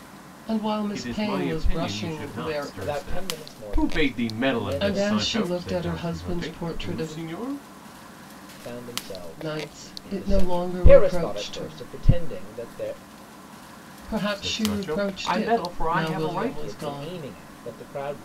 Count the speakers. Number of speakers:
three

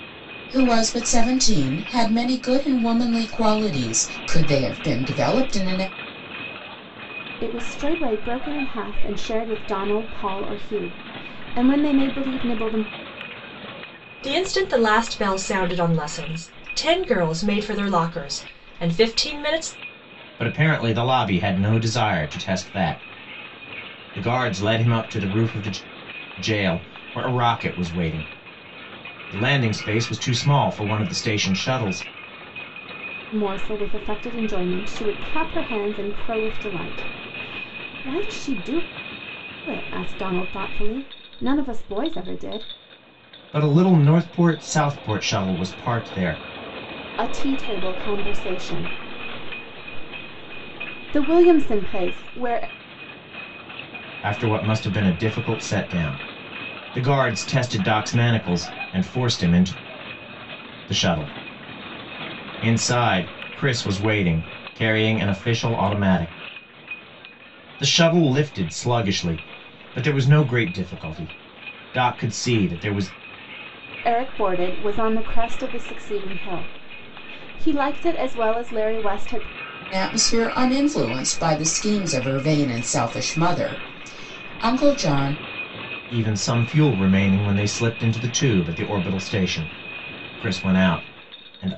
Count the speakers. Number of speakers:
four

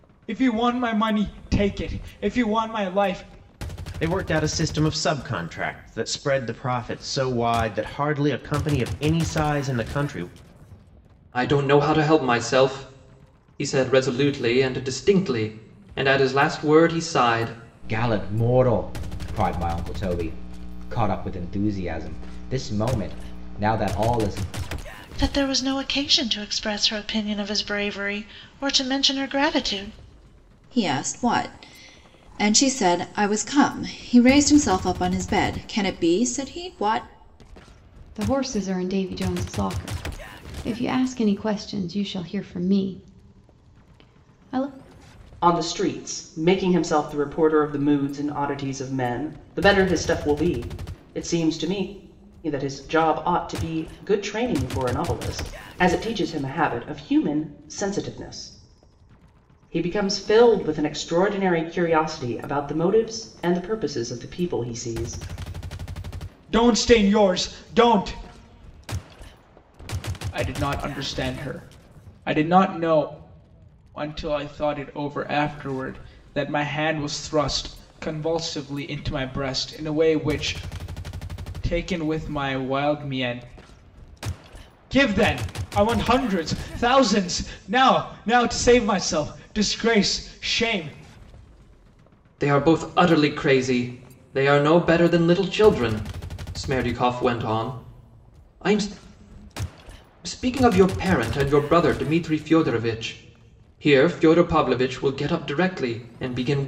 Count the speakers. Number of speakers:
eight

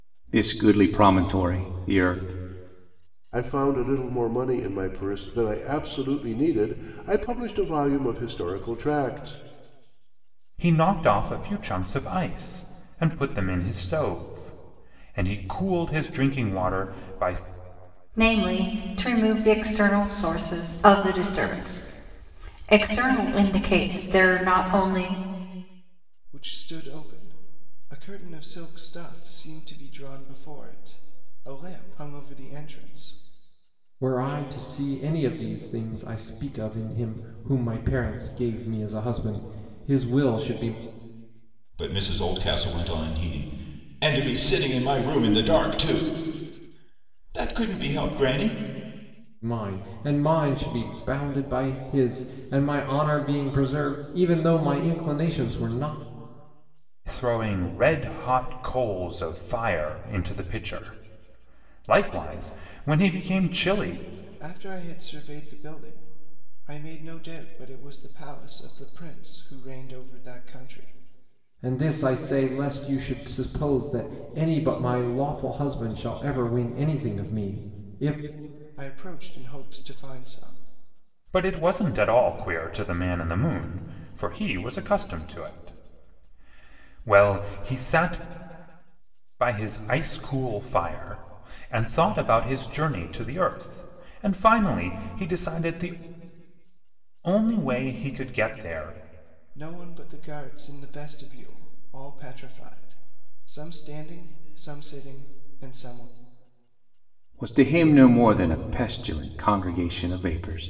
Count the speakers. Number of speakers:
seven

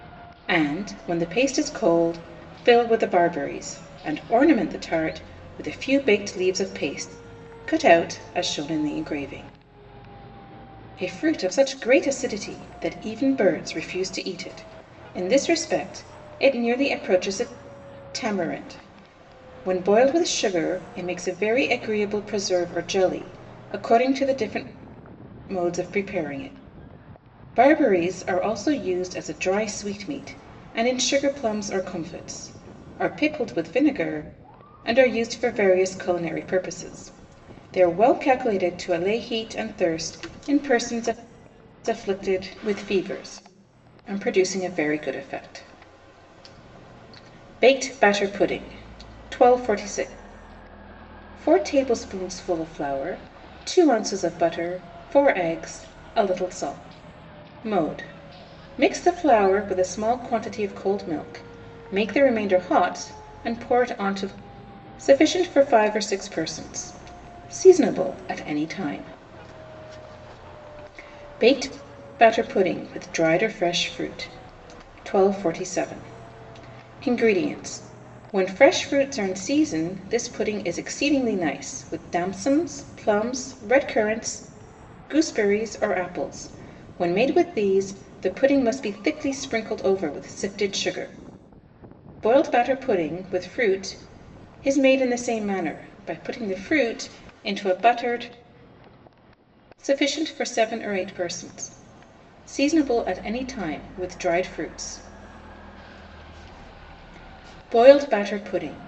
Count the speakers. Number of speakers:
one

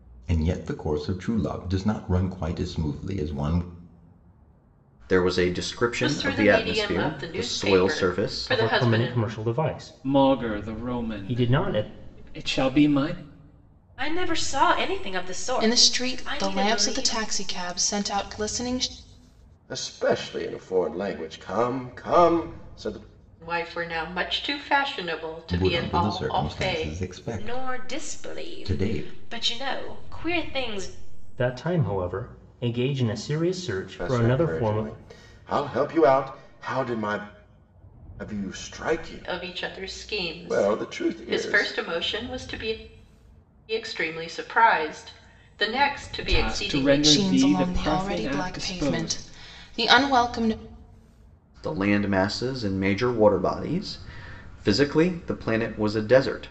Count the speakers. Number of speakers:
eight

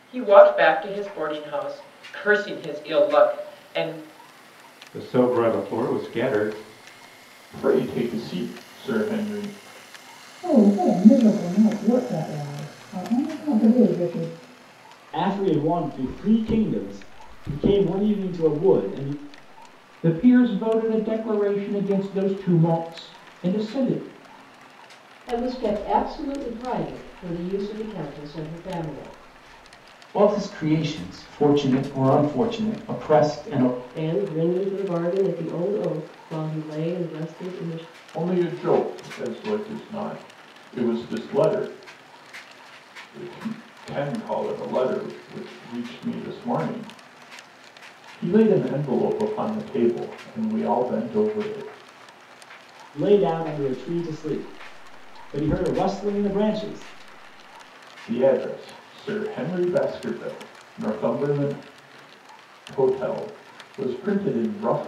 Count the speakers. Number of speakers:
nine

